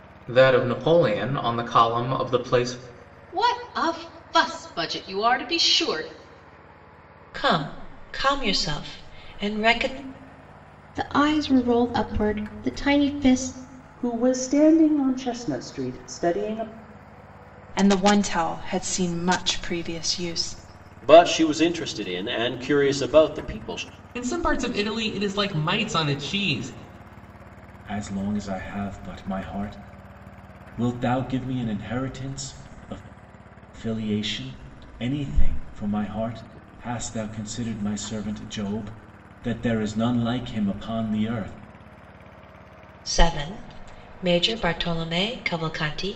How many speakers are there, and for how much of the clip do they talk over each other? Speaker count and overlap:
9, no overlap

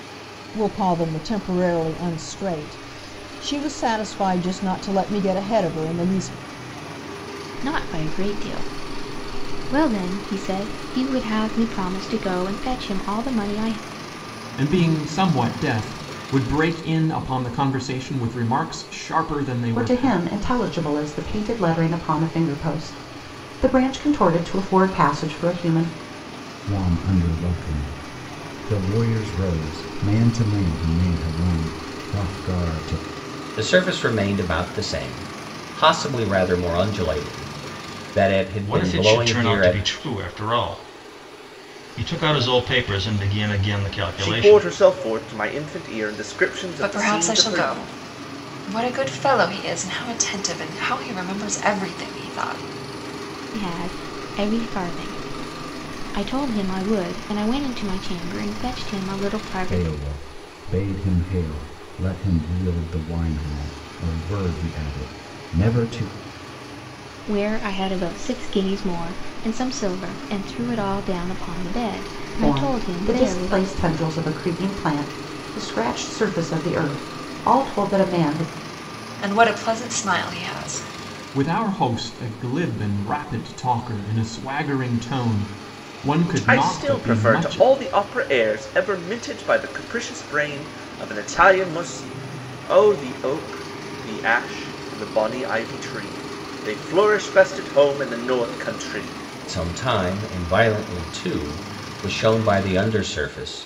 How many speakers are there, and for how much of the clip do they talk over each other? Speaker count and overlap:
9, about 7%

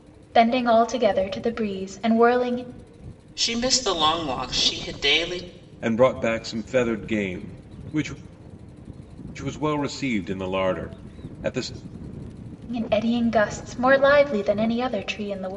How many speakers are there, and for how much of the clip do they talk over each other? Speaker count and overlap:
3, no overlap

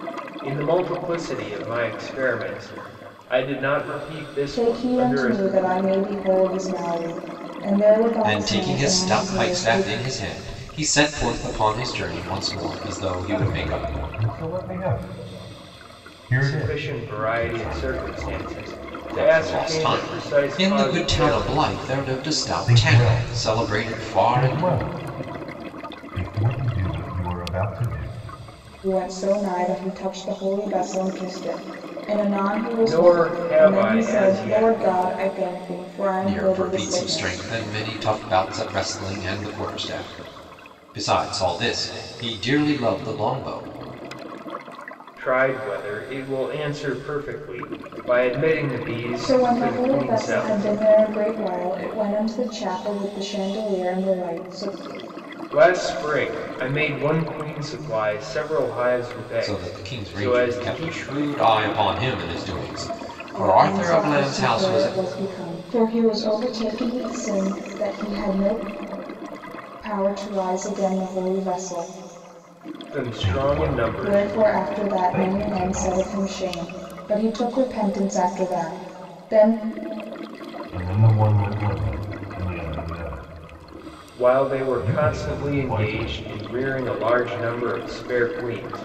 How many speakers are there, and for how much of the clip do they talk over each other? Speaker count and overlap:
4, about 26%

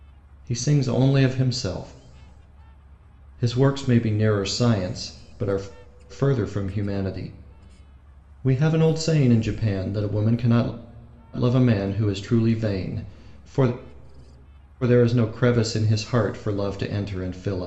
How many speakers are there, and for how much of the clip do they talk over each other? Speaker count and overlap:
1, no overlap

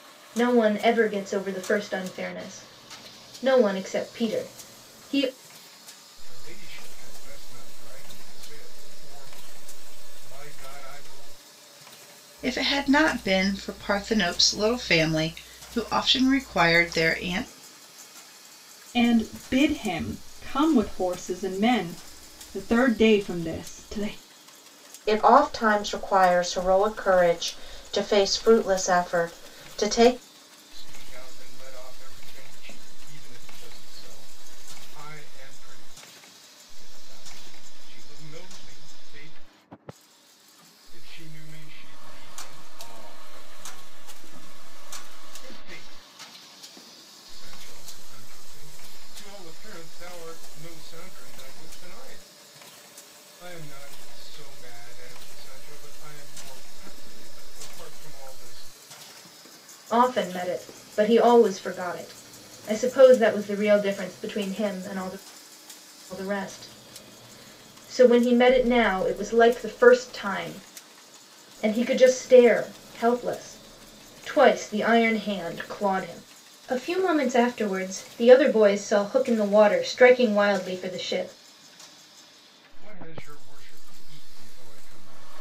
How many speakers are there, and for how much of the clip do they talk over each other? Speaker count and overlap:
5, no overlap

